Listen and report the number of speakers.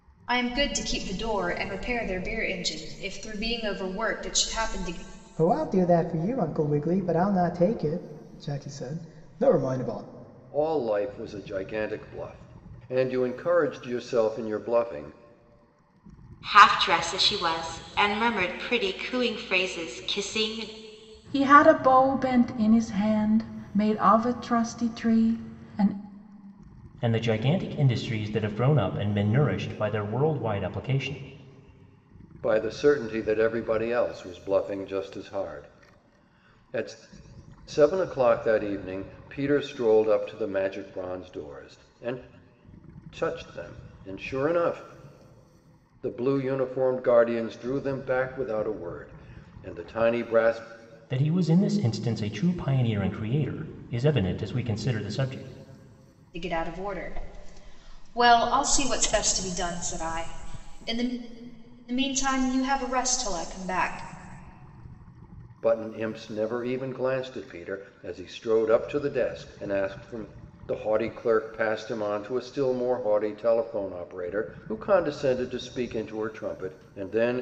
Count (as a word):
six